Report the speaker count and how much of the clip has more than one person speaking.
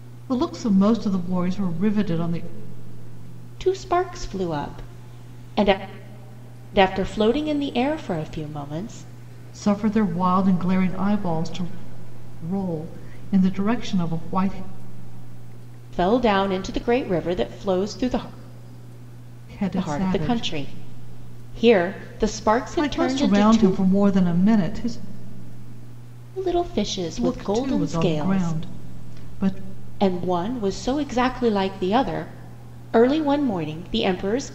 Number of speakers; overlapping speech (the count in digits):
2, about 9%